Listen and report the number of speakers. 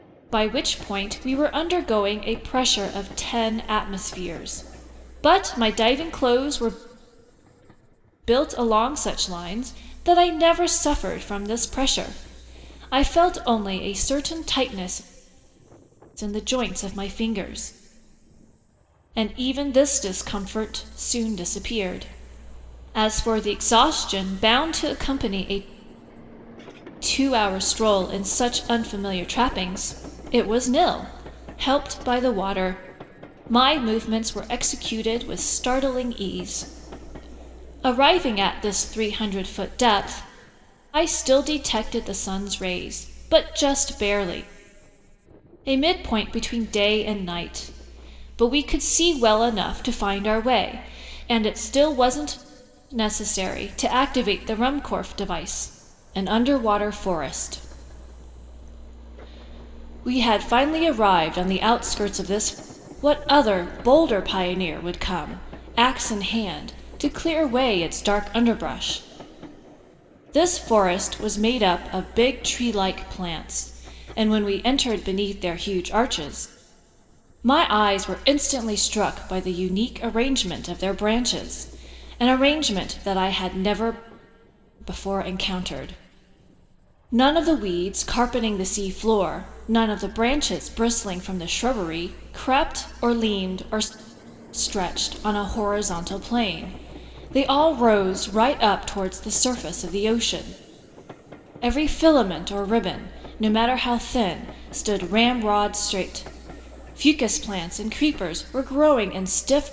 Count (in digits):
1